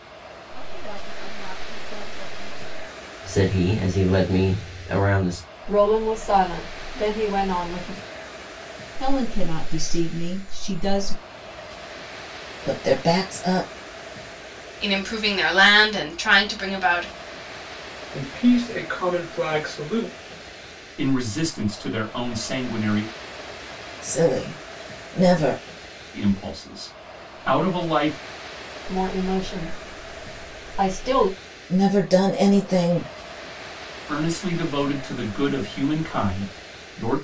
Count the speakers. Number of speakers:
eight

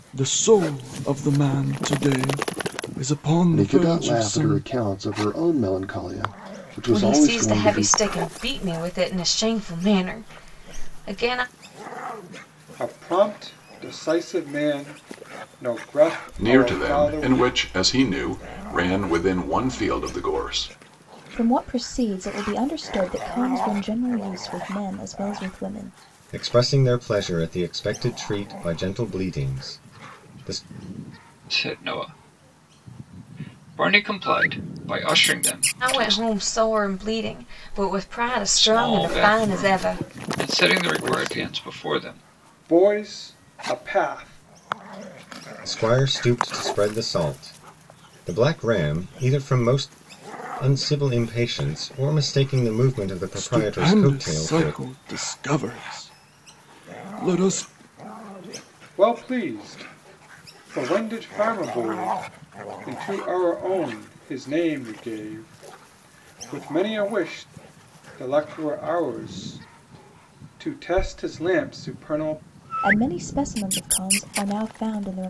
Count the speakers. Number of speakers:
eight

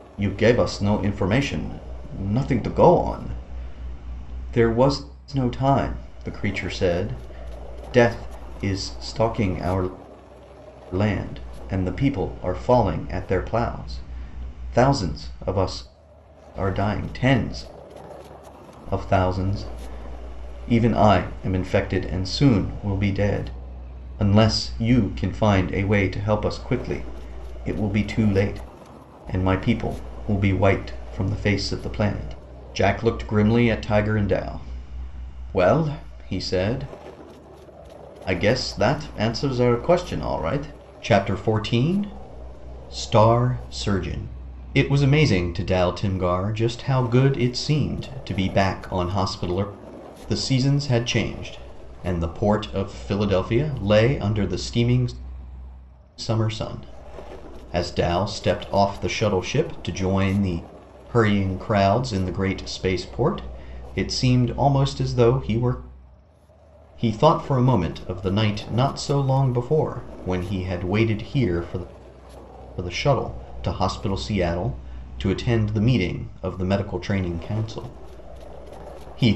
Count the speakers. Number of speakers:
one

